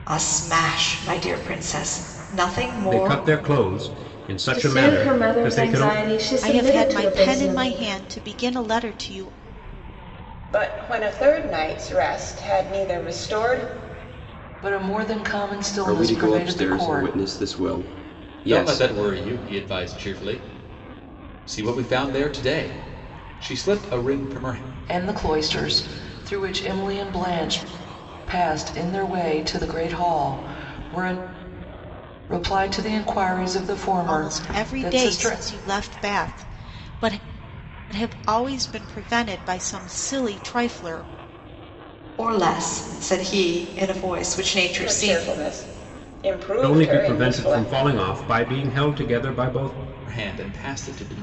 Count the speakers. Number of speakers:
8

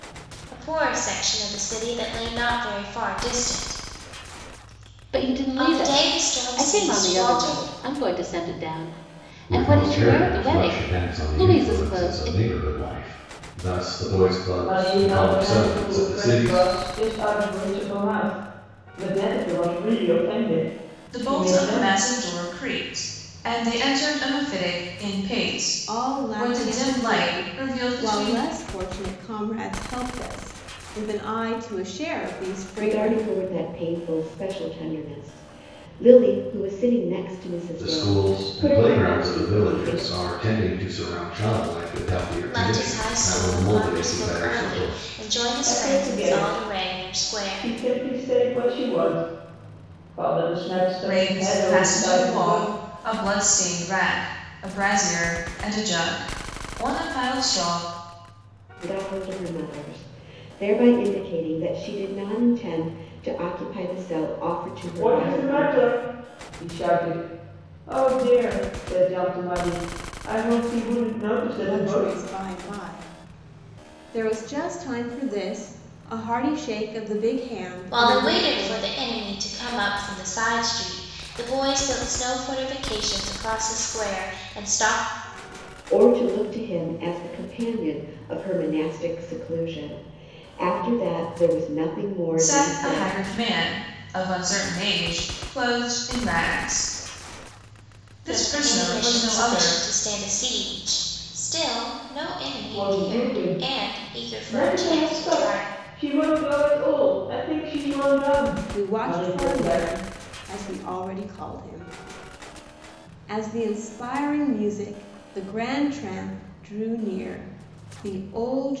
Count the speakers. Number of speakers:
7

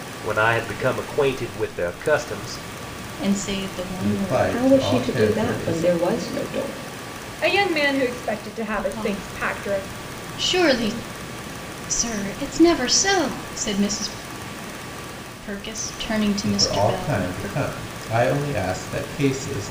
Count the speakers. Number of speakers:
5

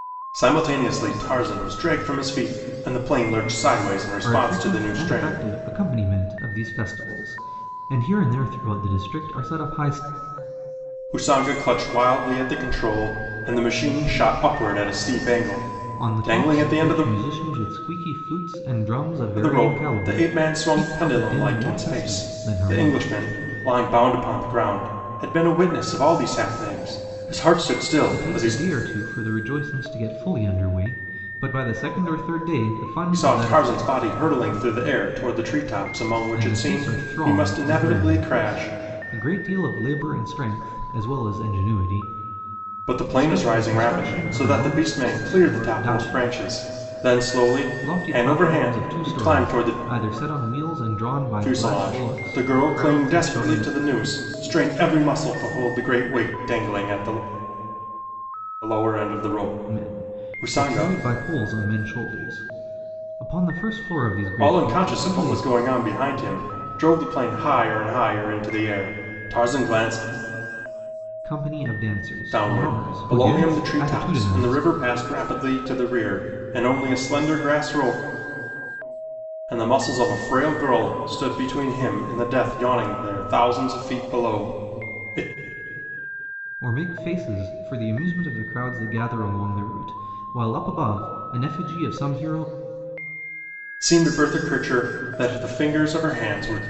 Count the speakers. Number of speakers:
2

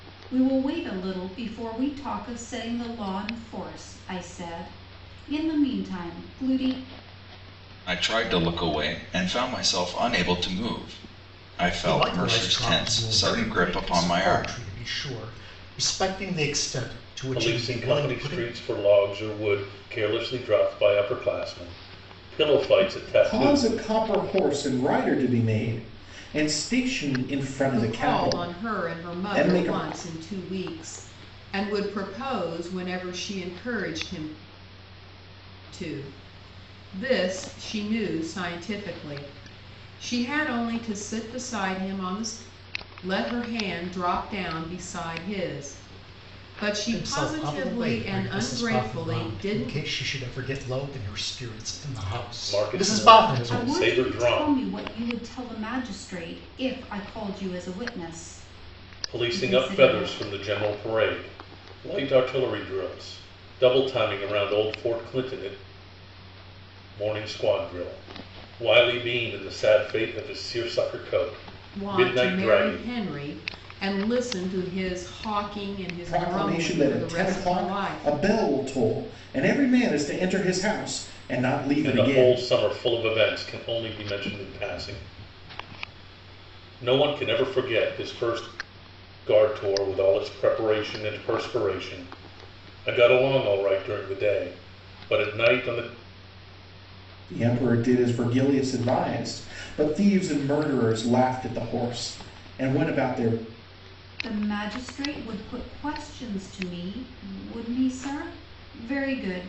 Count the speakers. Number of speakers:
6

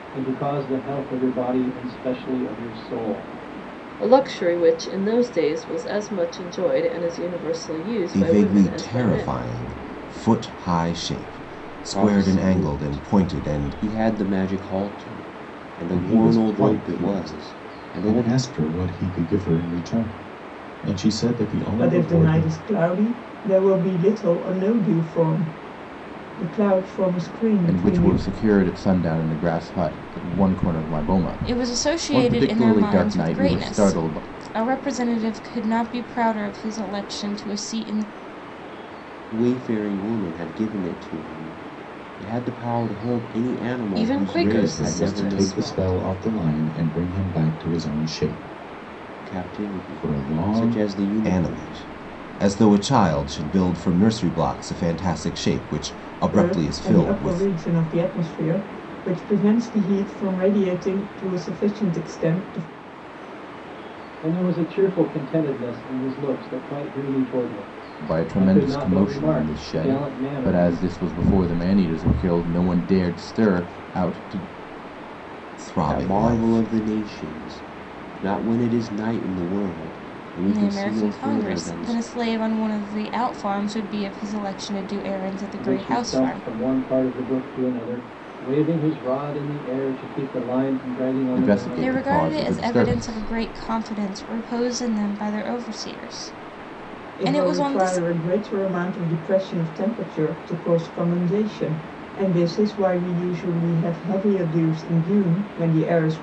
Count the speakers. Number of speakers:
8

